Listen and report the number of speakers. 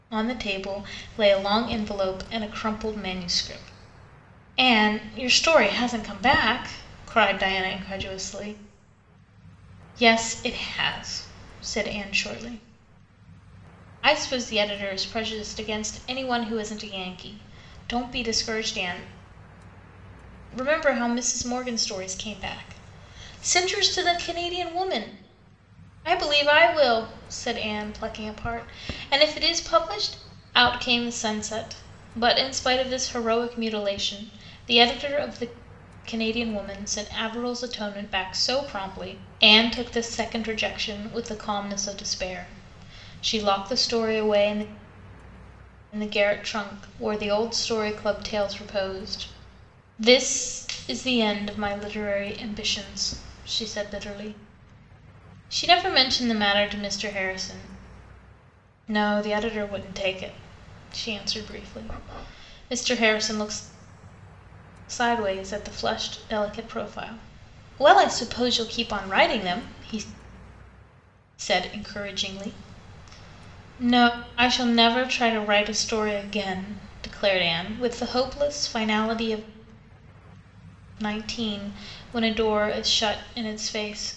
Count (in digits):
1